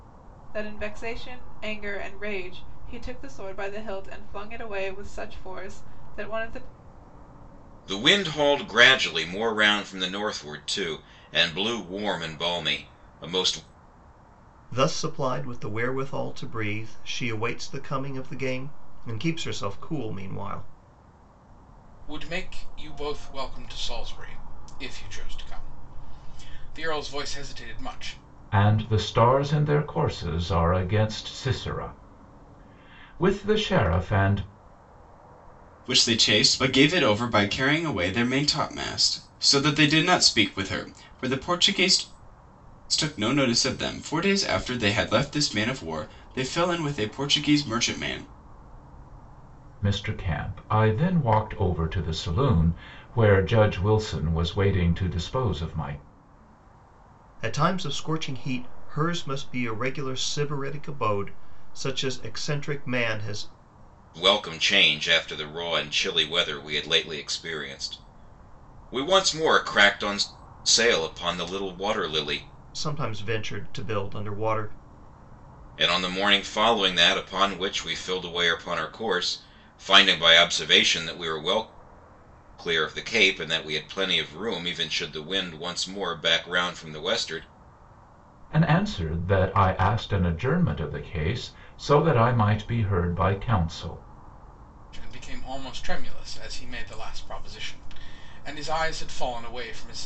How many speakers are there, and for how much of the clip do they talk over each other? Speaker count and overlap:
6, no overlap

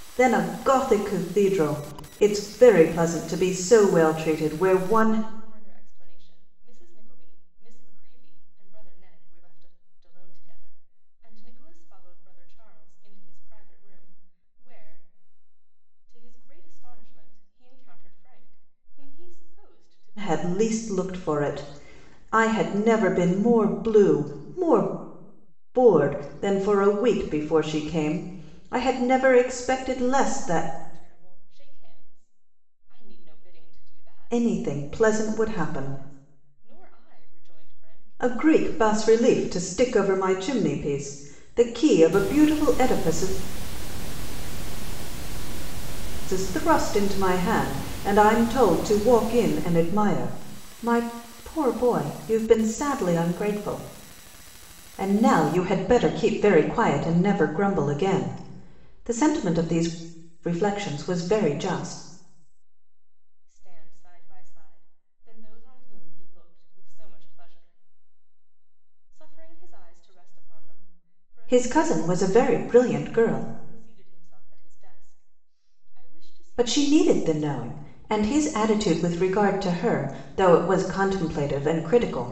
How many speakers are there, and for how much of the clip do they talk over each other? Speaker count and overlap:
2, about 12%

